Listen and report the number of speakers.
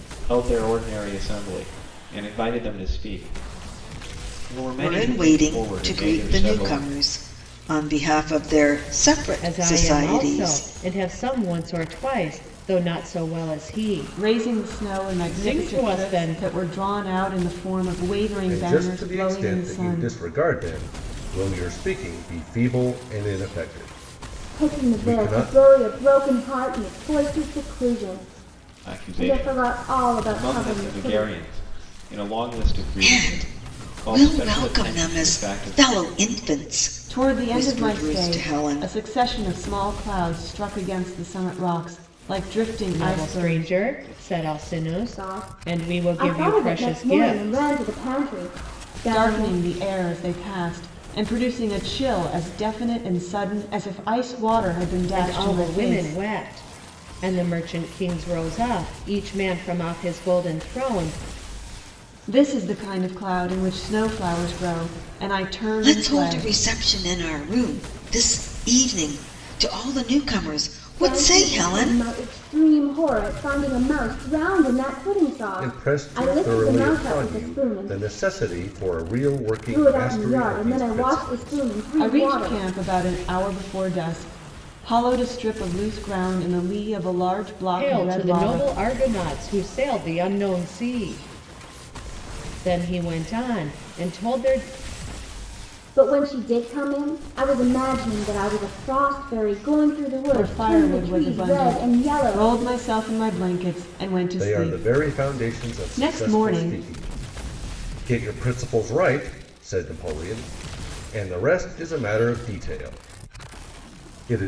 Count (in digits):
6